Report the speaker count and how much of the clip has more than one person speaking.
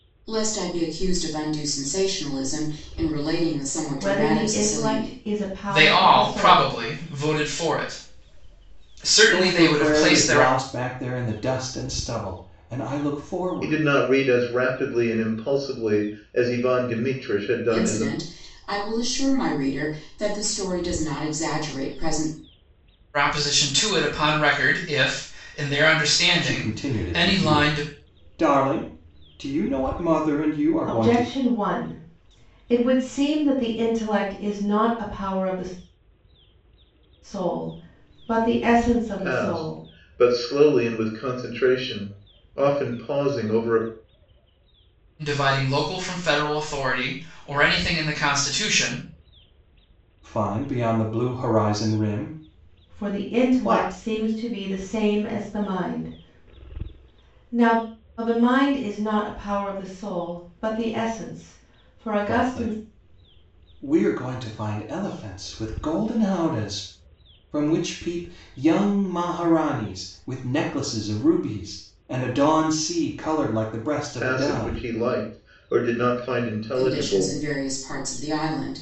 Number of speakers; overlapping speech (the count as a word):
five, about 13%